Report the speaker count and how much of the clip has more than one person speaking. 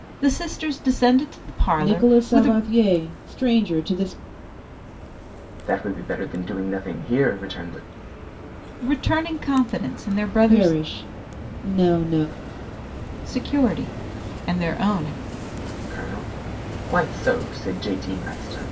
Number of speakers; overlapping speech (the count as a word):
three, about 6%